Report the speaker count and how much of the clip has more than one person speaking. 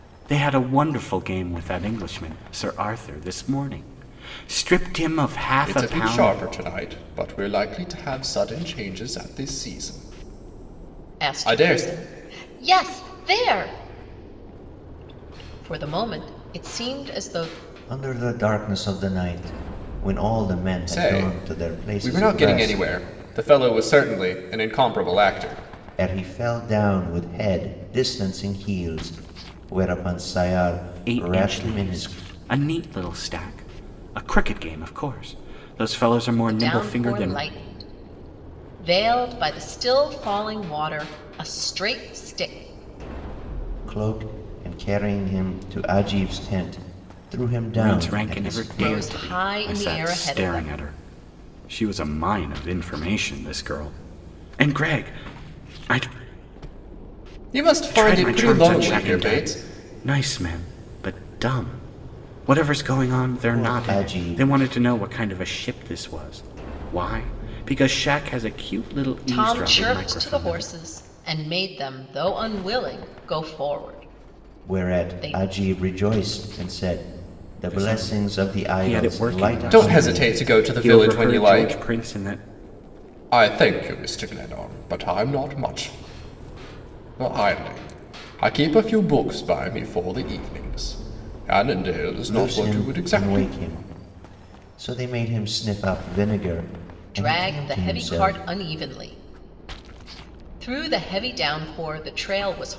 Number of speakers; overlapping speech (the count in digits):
4, about 20%